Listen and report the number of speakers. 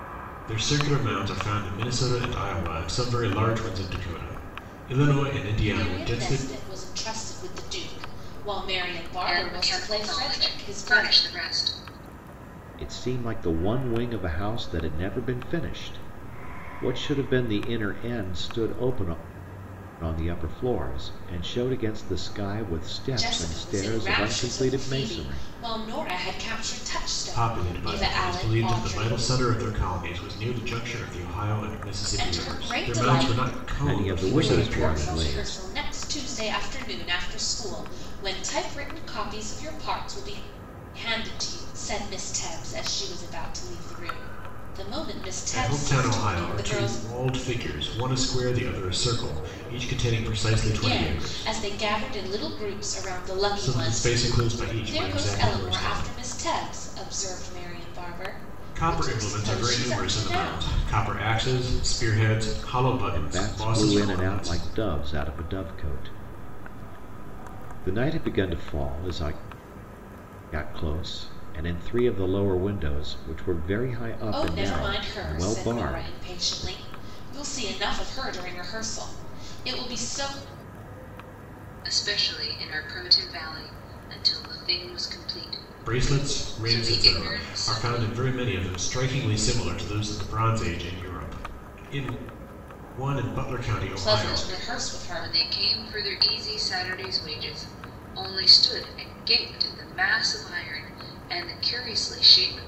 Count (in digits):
4